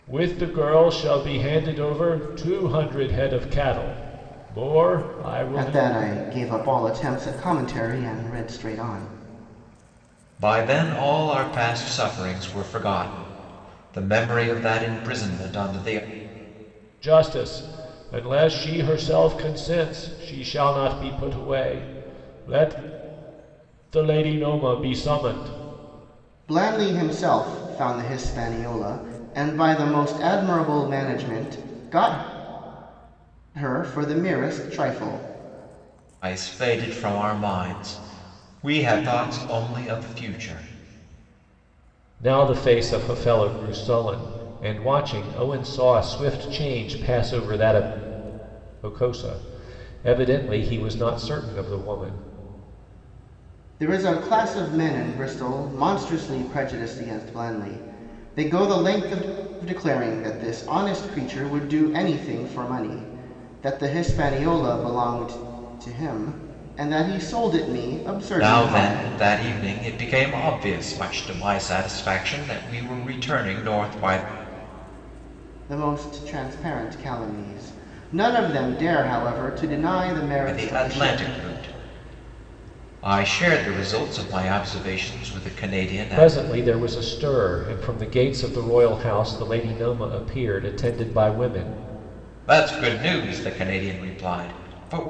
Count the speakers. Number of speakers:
3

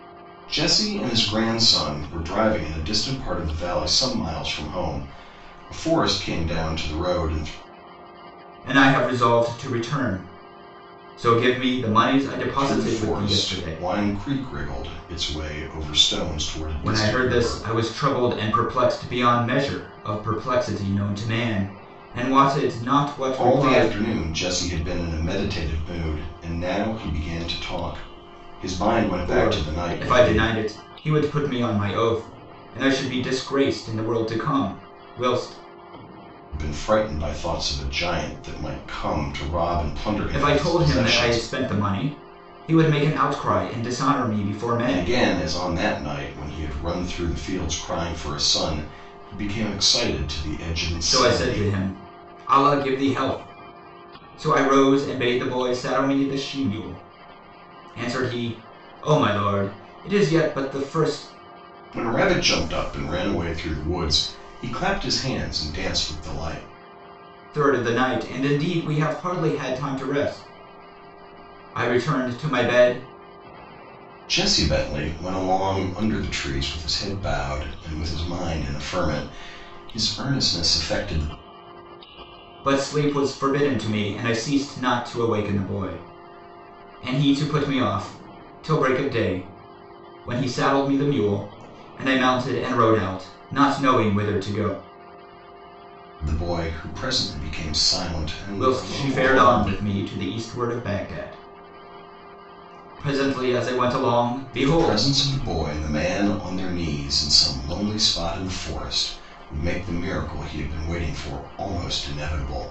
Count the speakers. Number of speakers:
2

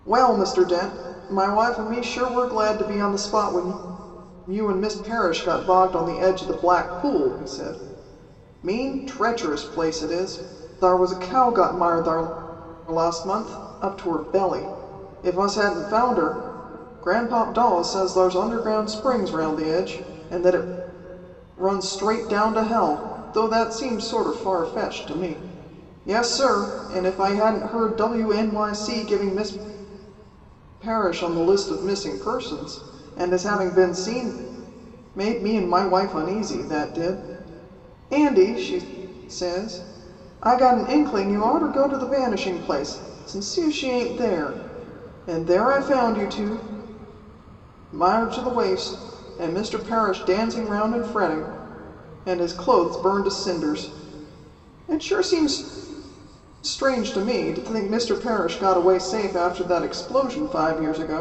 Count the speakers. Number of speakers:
1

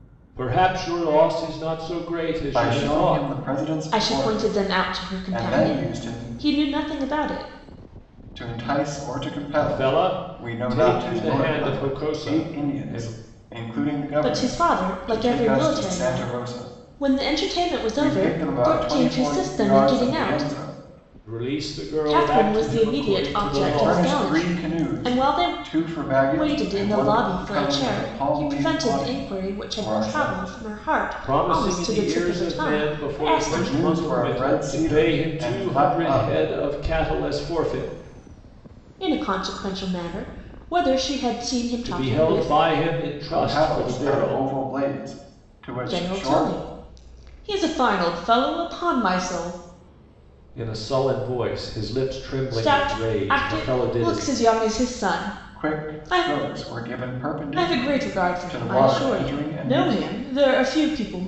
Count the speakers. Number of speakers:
3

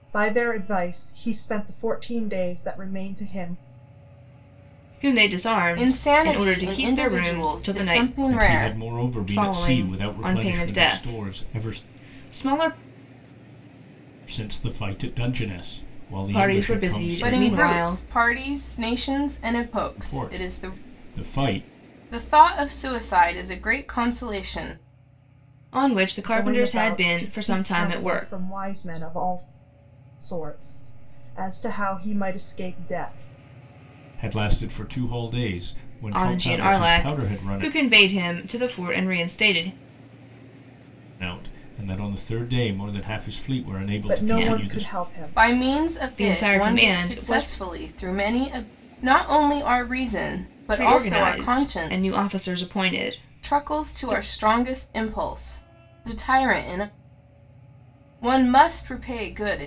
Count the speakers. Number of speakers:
4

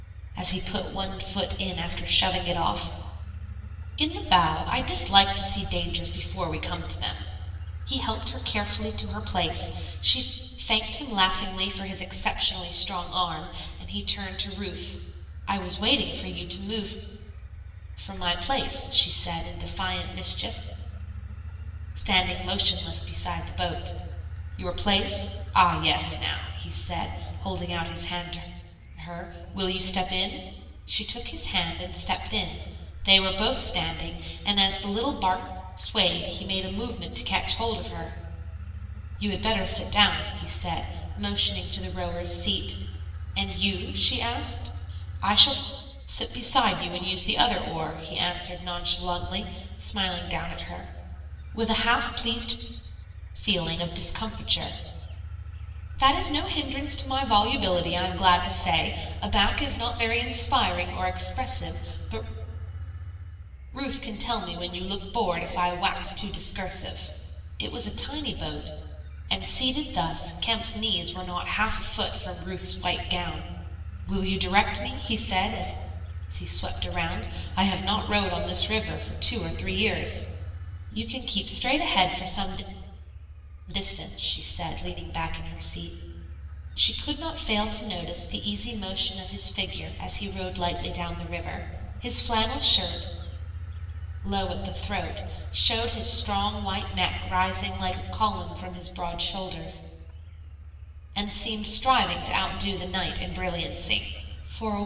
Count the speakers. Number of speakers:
1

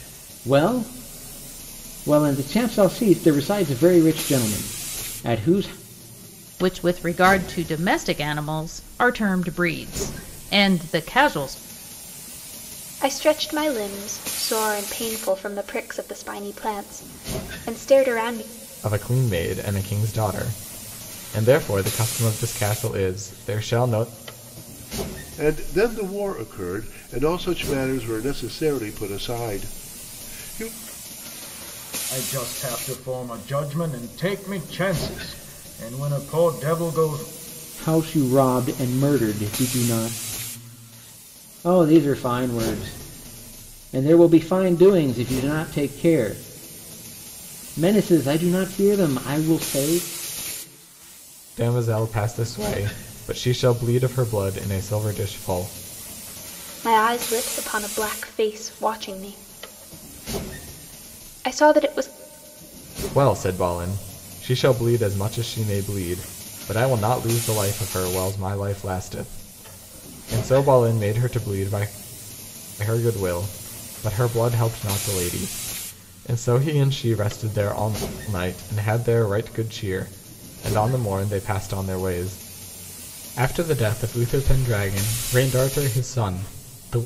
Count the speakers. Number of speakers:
6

